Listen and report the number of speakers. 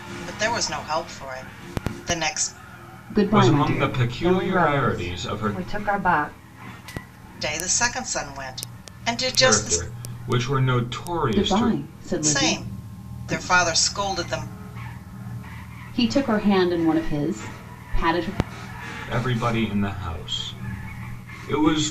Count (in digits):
4